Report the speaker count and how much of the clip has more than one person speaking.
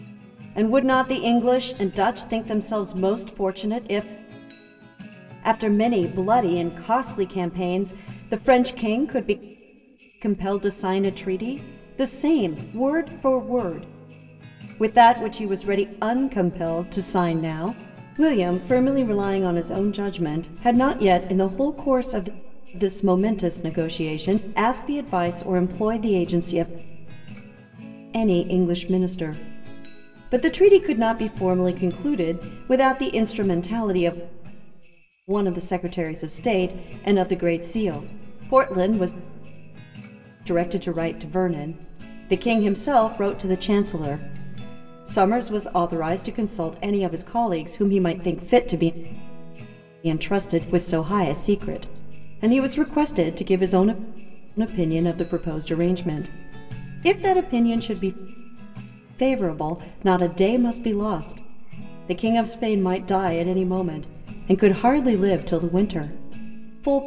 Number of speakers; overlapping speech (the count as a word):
one, no overlap